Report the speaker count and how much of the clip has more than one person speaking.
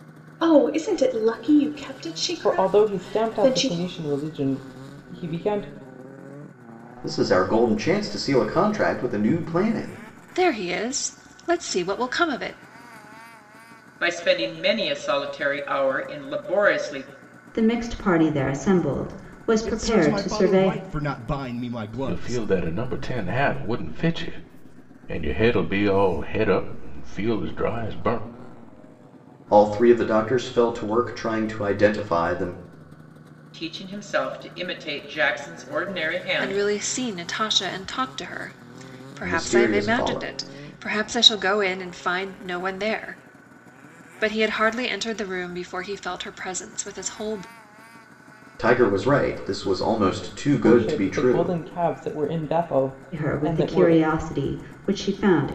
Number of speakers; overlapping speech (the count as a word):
eight, about 11%